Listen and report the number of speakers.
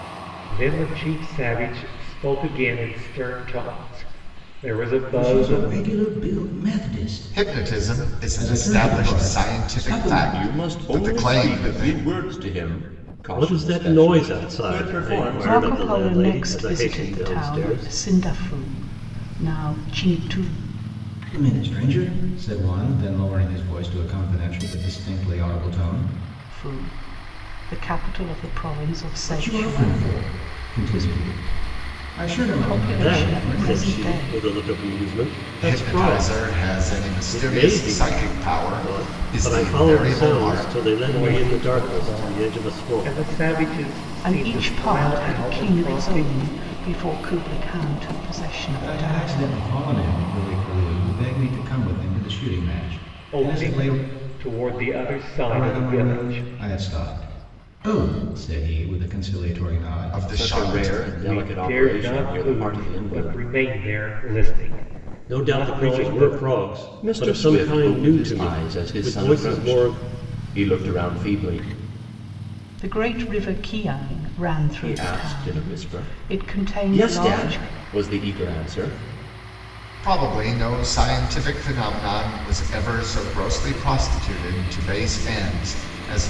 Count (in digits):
6